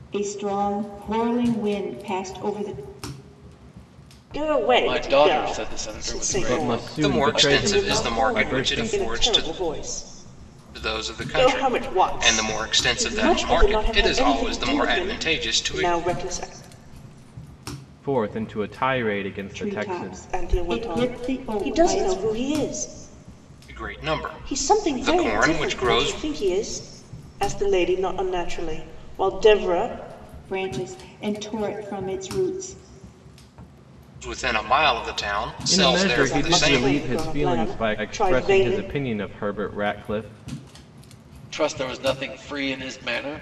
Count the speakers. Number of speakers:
five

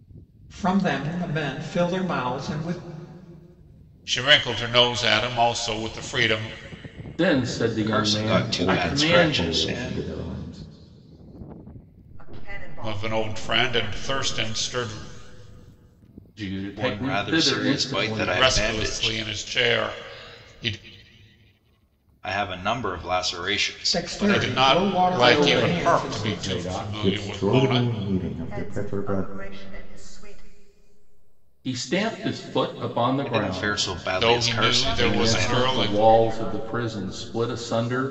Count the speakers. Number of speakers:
six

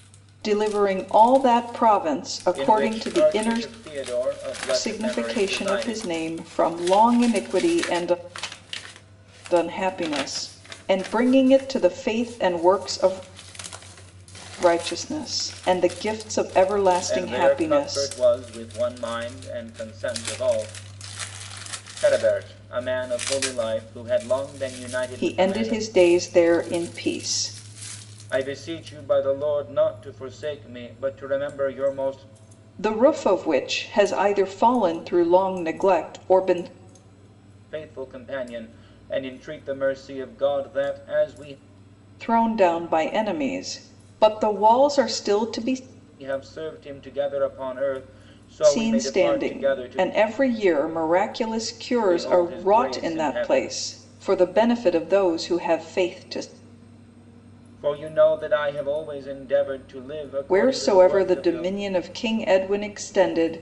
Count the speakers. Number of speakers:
two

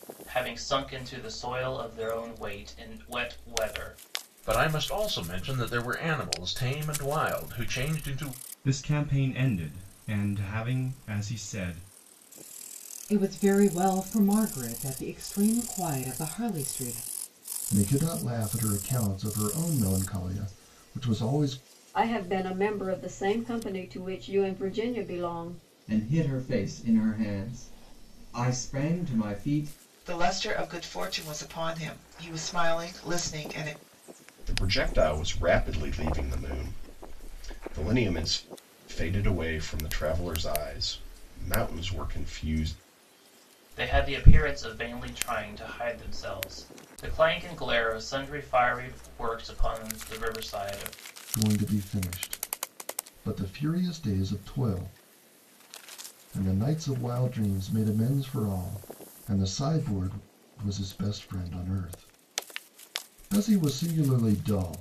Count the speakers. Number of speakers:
nine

